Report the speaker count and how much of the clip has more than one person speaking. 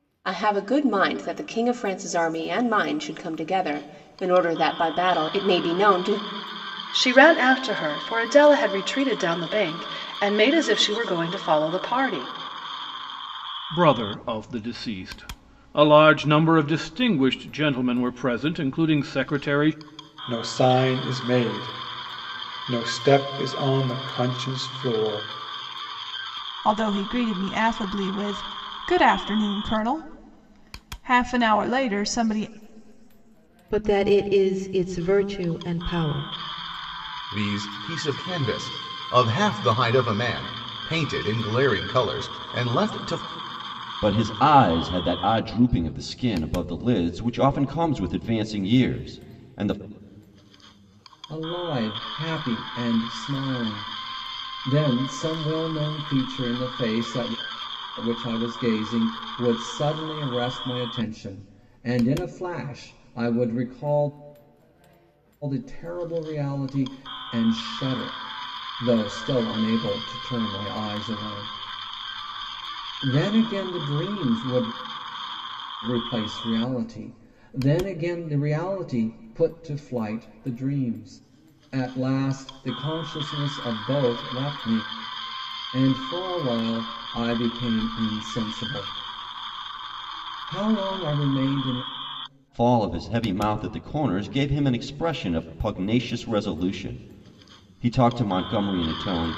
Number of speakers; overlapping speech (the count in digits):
9, no overlap